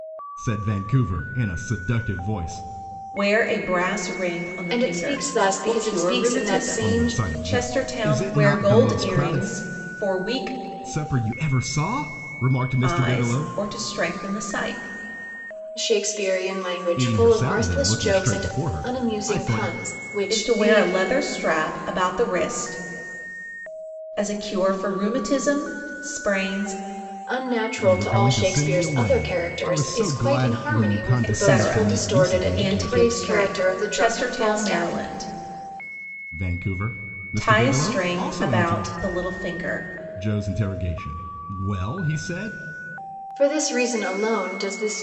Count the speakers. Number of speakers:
three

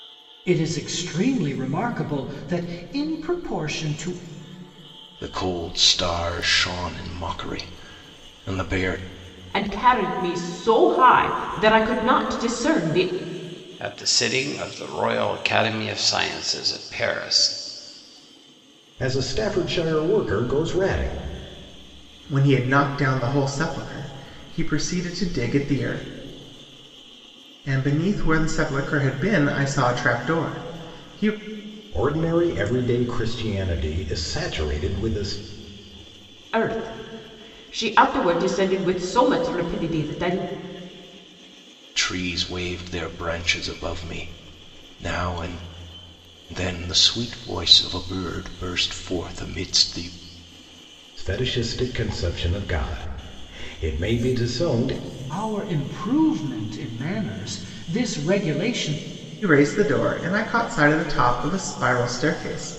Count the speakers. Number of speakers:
six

